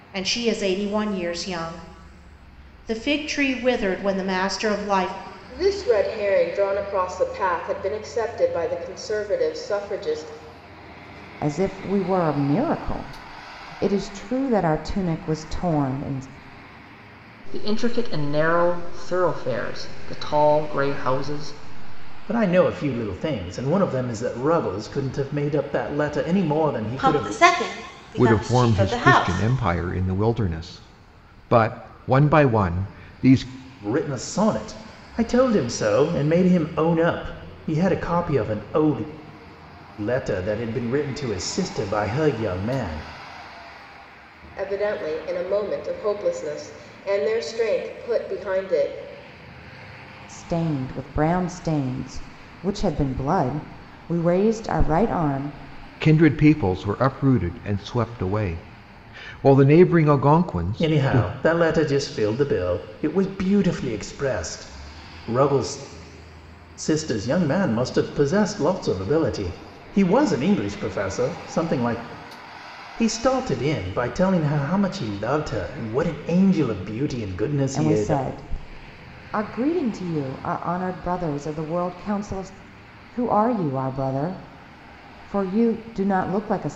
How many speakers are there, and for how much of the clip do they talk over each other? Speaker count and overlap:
7, about 3%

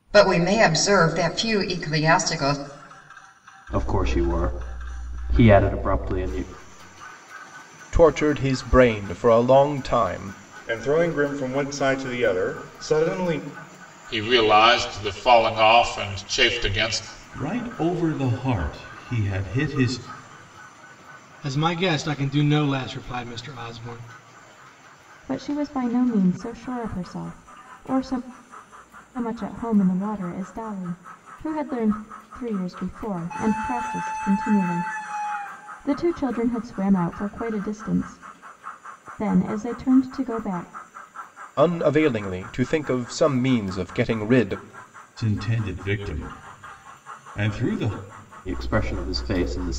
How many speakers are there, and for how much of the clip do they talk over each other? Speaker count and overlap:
8, no overlap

